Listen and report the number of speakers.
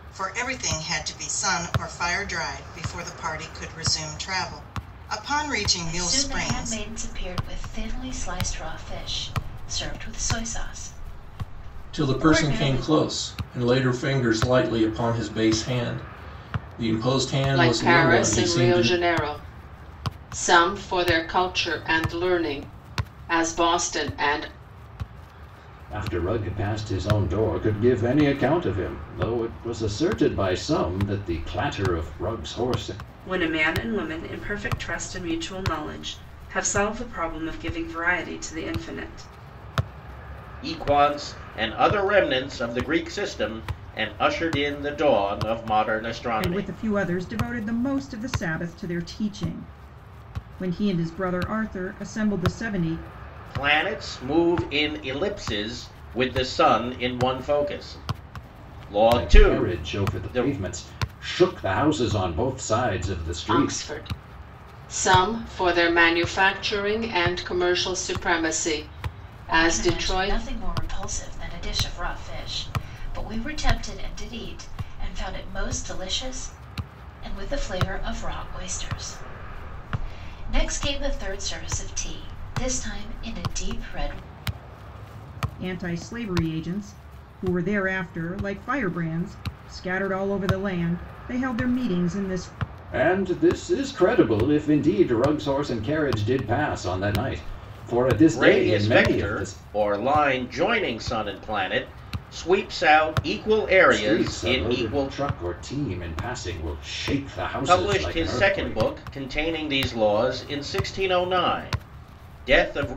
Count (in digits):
8